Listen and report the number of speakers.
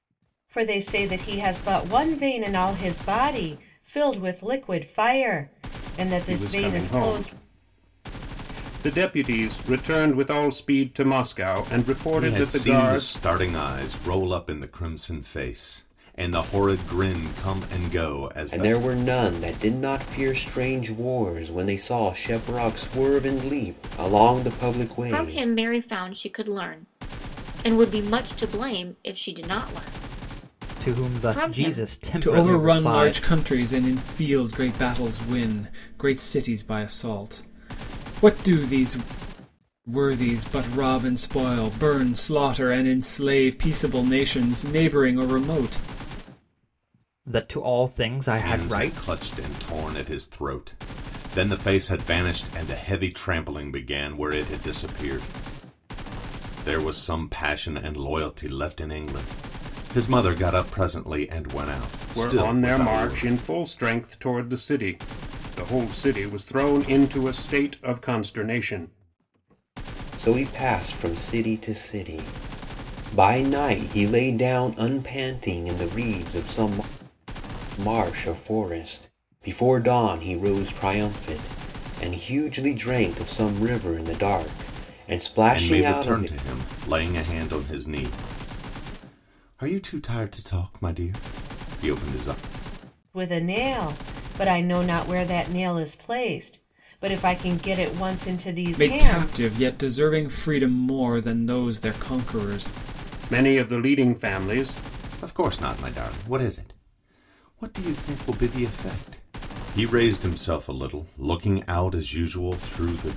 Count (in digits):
7